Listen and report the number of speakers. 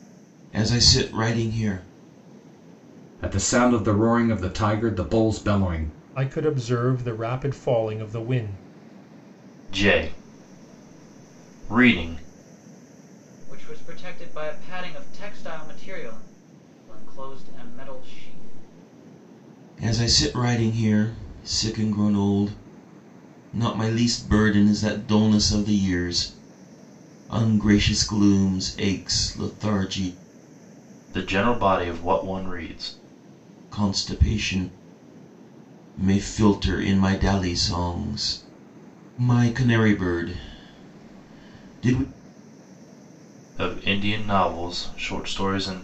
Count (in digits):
5